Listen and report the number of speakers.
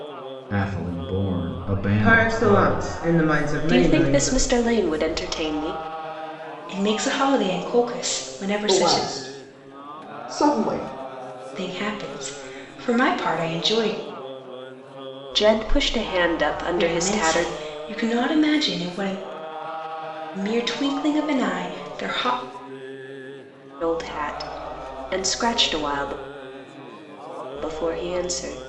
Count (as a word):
five